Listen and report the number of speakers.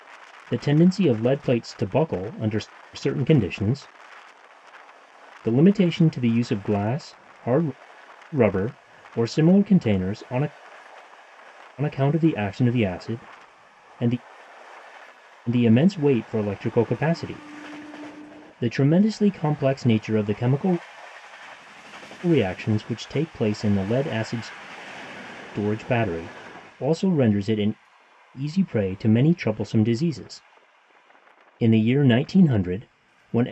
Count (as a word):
one